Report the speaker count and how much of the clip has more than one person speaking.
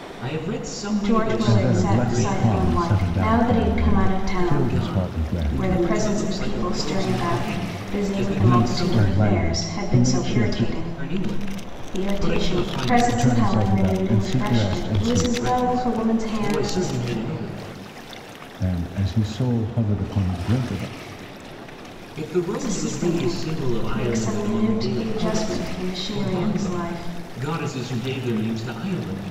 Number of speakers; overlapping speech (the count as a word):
three, about 67%